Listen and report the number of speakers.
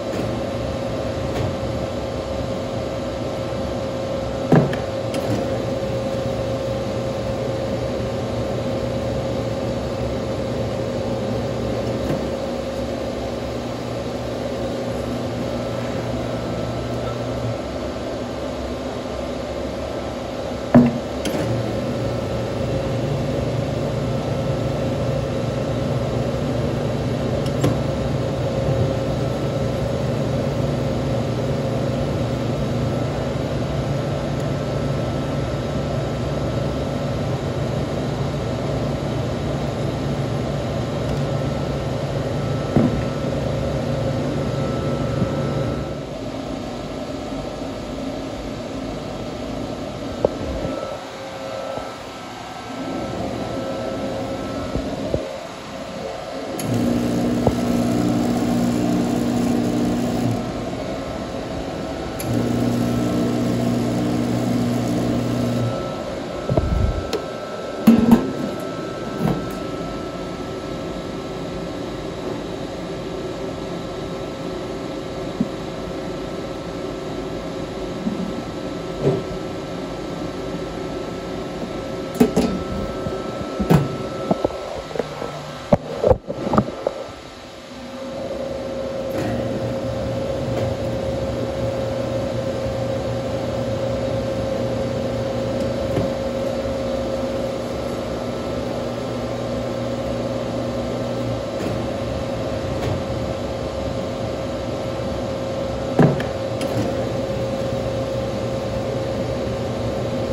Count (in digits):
0